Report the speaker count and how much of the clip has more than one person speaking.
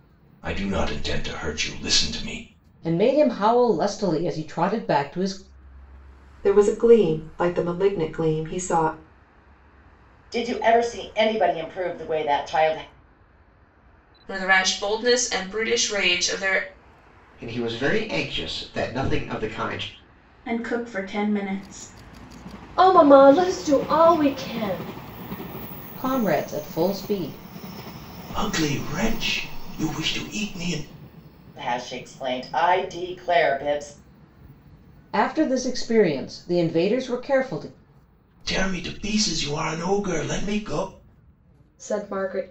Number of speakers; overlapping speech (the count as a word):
eight, no overlap